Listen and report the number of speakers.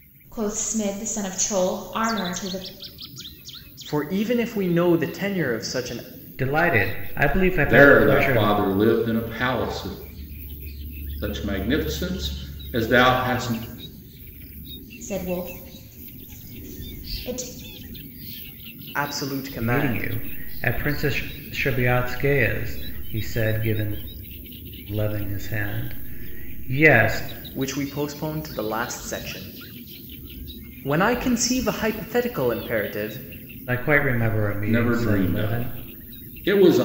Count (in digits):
4